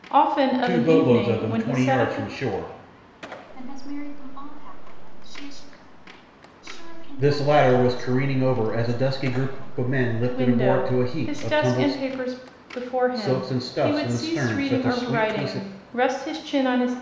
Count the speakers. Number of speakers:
three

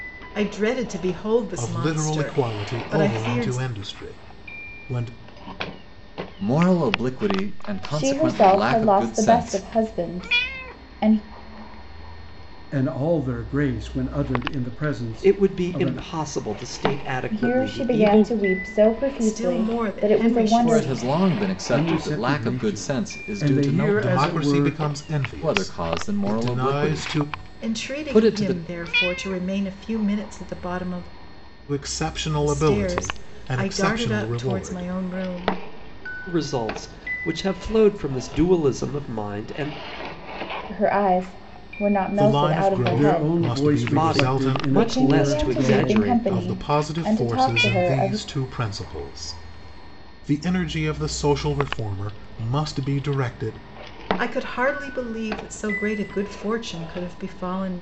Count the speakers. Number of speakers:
six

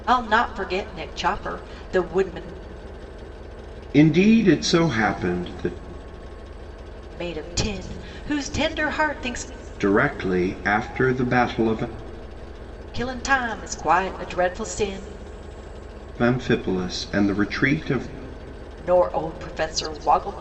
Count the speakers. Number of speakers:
two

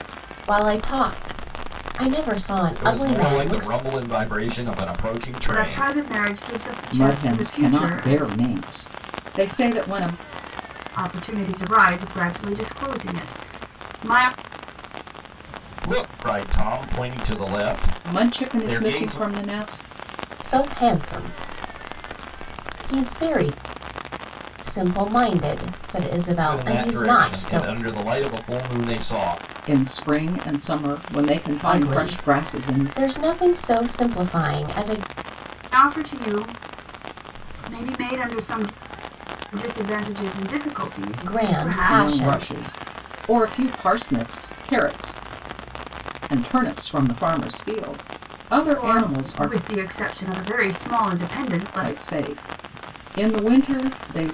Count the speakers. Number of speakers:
four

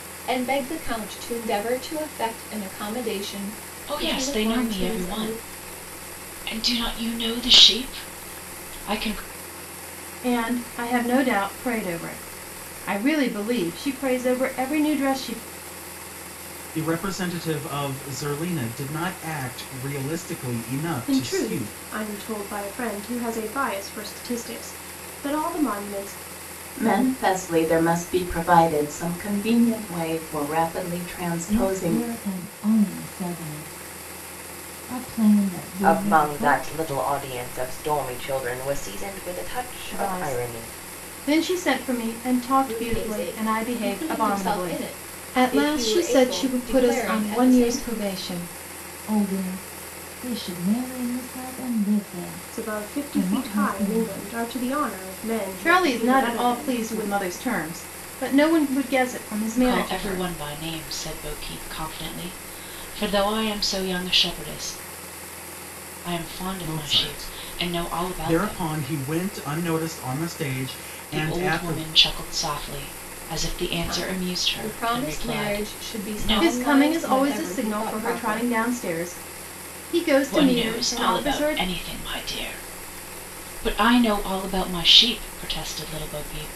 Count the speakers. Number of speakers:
eight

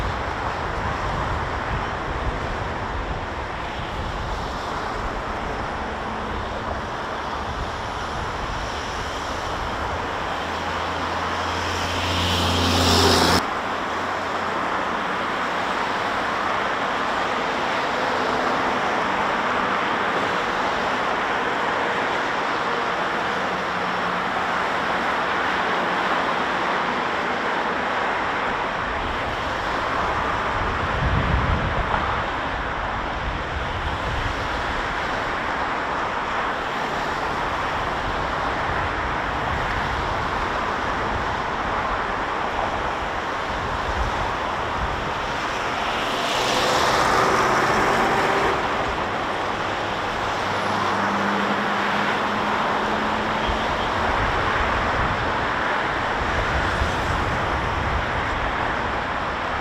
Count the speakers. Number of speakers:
zero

